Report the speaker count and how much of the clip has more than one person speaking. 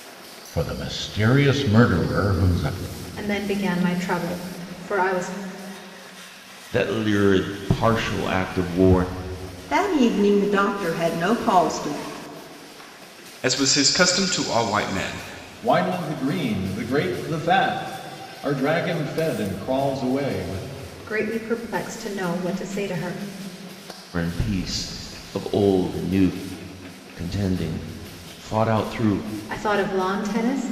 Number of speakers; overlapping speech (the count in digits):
6, no overlap